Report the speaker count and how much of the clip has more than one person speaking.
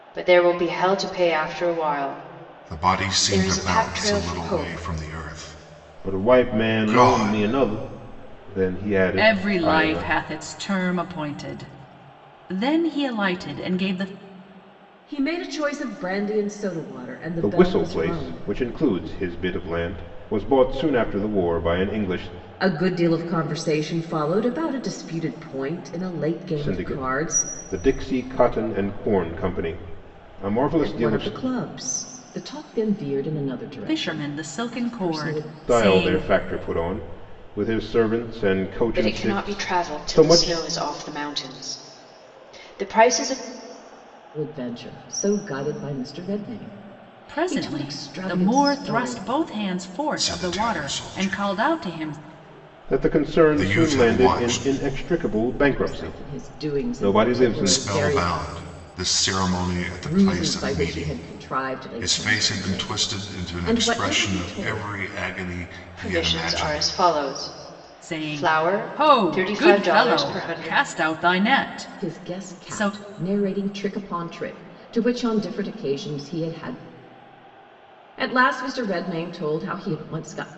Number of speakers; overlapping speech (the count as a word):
five, about 36%